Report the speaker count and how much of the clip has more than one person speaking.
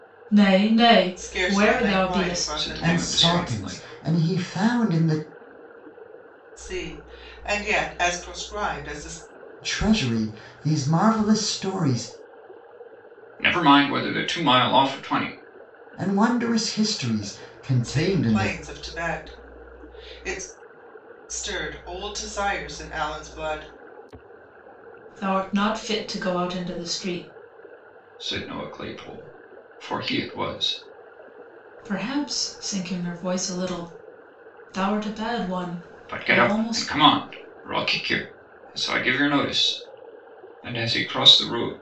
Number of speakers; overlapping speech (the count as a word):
four, about 10%